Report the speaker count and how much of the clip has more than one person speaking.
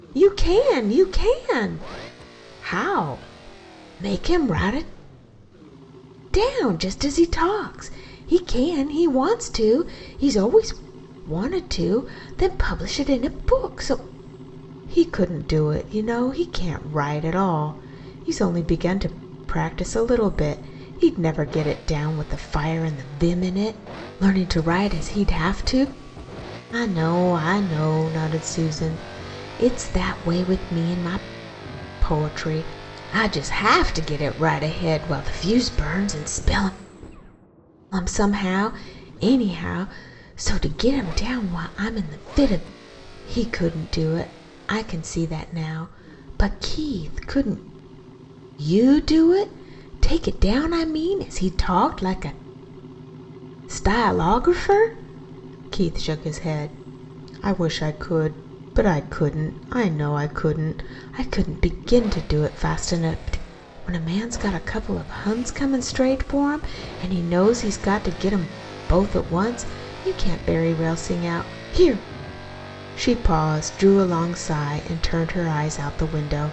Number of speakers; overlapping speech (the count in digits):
1, no overlap